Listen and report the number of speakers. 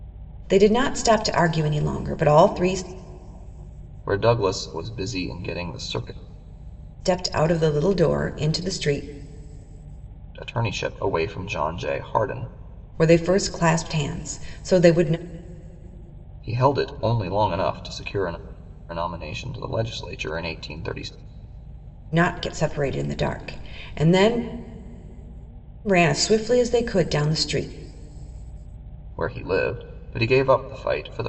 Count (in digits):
2